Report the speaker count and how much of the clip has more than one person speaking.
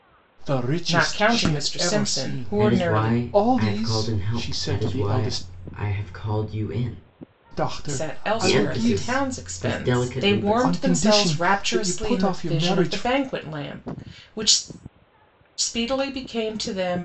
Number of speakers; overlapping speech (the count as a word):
three, about 57%